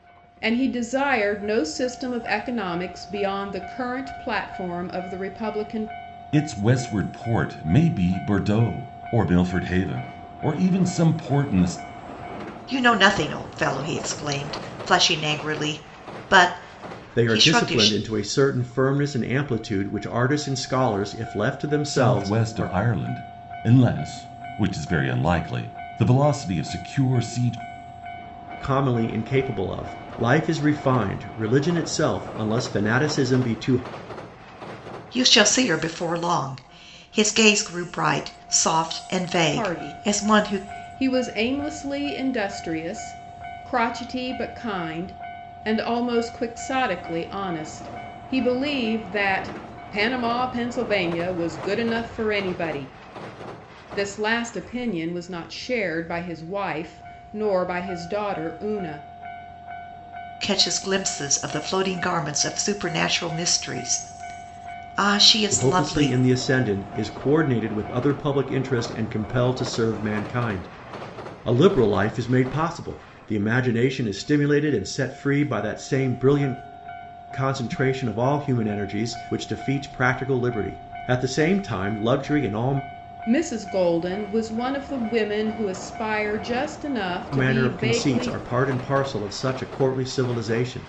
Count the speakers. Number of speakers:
4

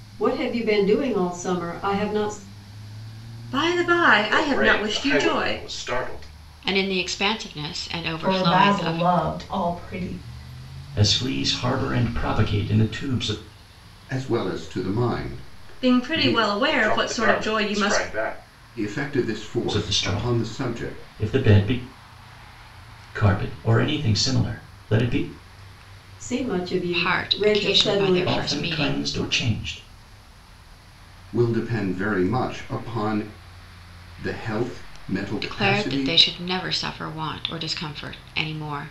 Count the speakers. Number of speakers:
7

